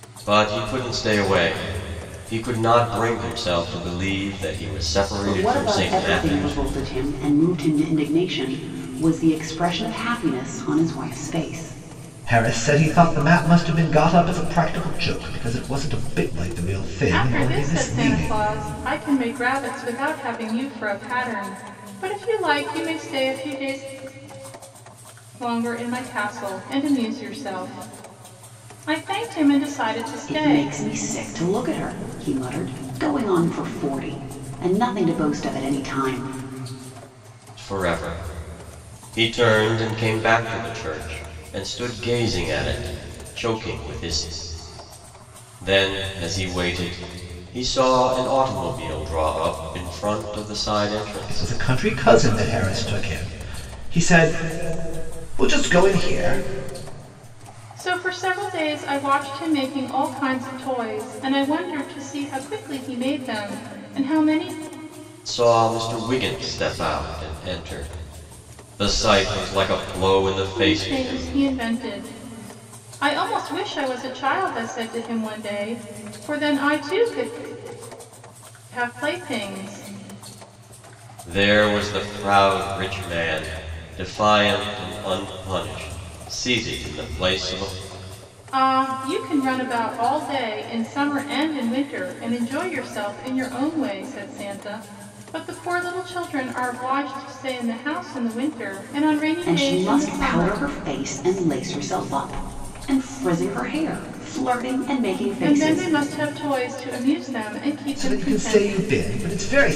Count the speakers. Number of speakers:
4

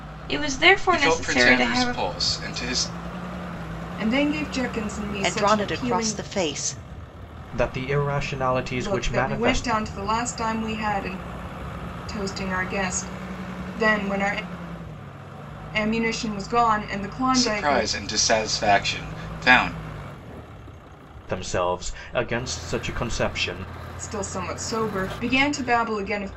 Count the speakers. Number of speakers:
5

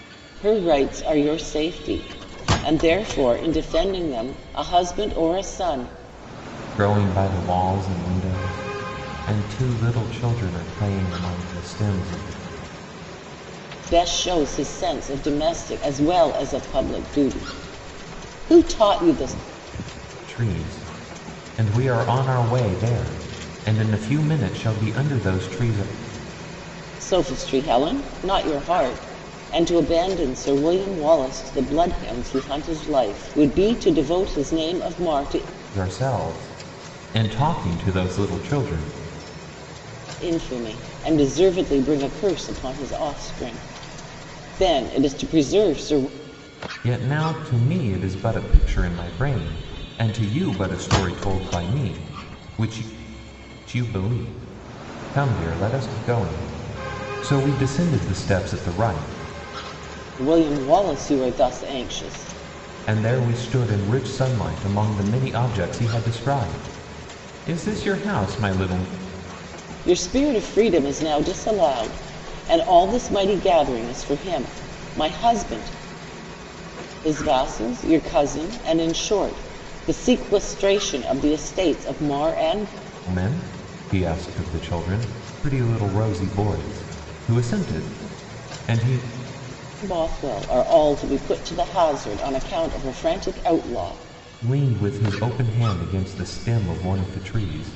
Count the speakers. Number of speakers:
2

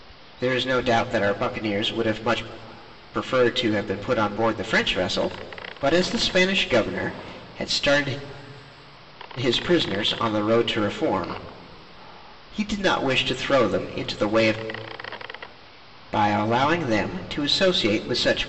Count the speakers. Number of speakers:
1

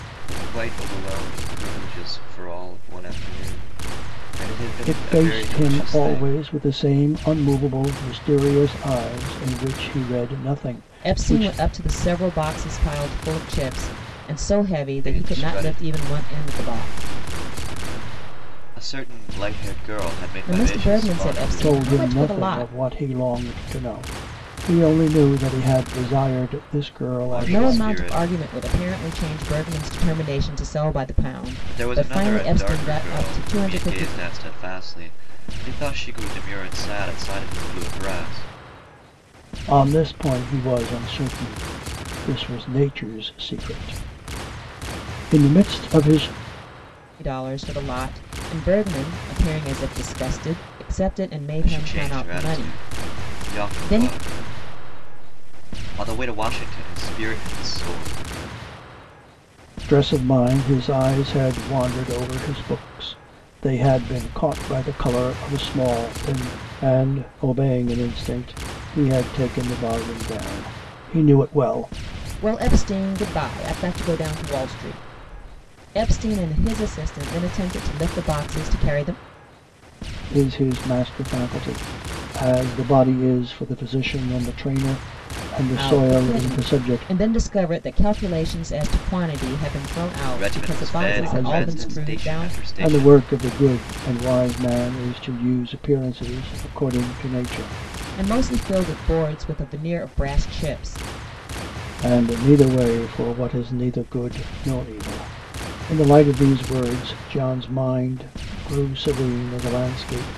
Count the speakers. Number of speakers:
3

